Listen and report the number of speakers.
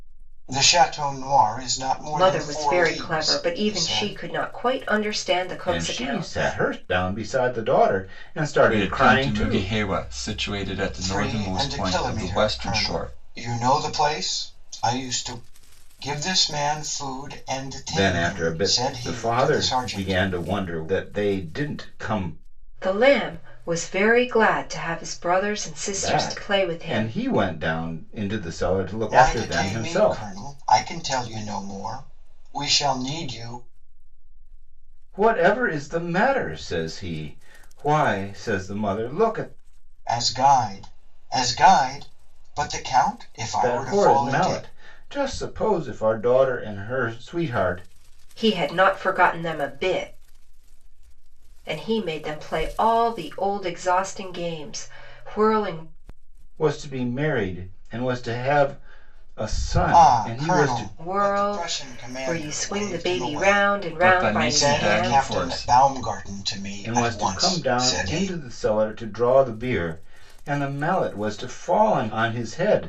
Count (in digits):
4